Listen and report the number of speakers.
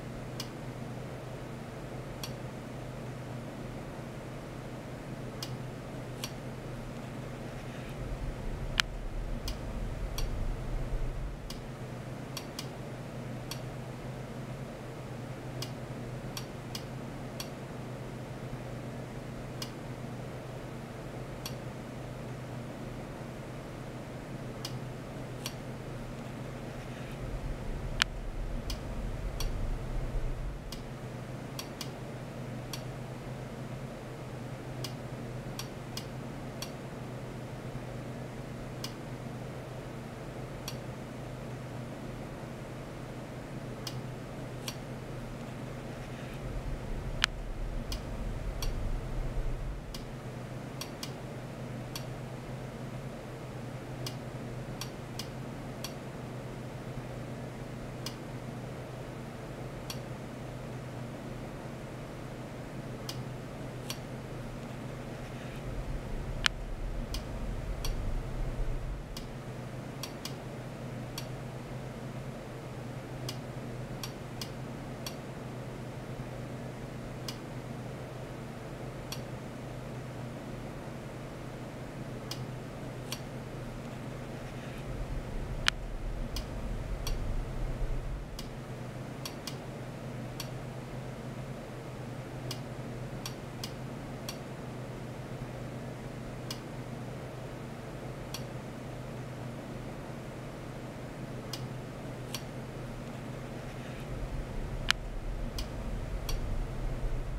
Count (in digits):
0